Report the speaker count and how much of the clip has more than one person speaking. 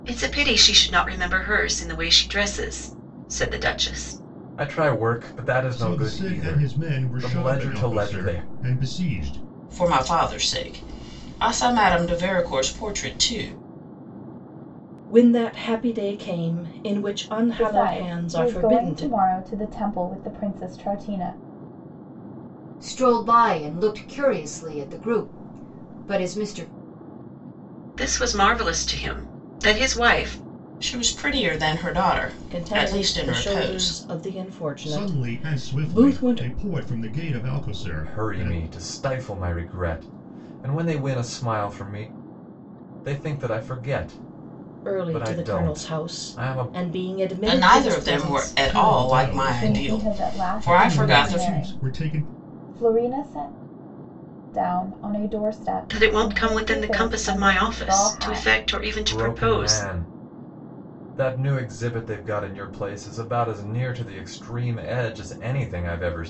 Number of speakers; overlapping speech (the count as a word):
seven, about 28%